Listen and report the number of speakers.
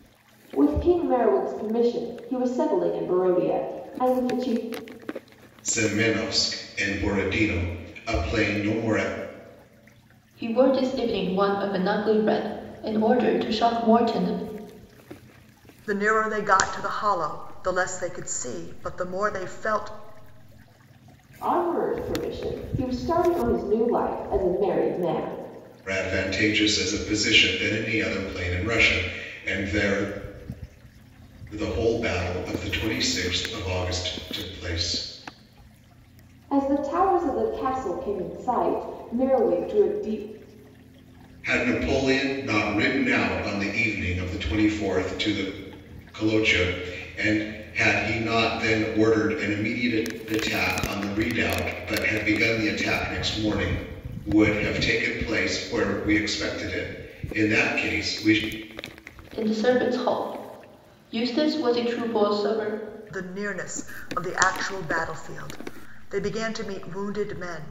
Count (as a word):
four